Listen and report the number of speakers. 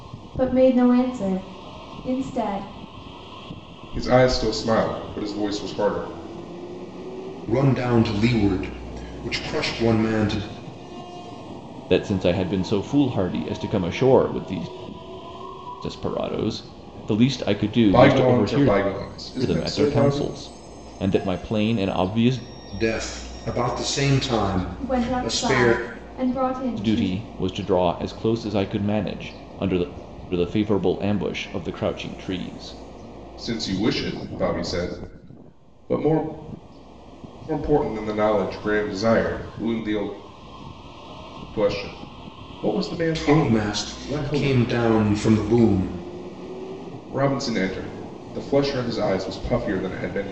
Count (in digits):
4